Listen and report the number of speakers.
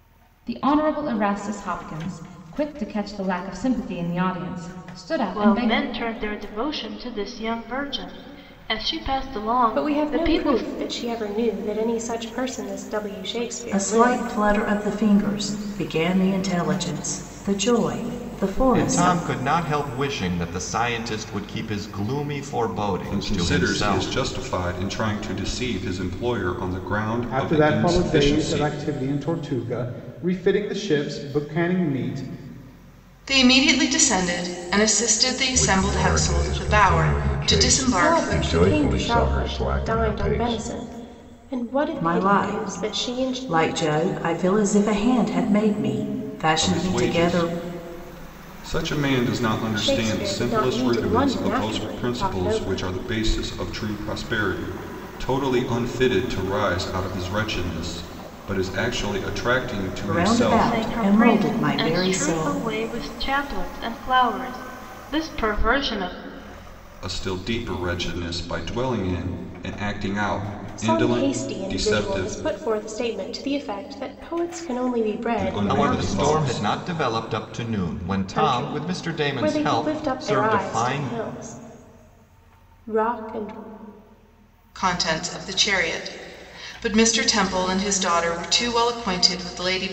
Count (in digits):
9